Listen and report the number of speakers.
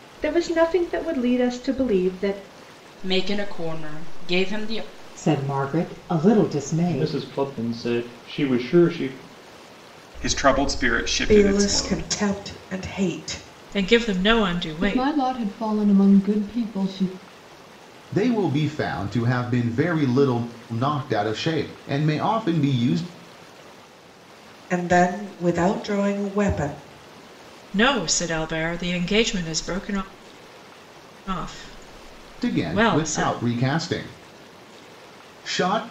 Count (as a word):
nine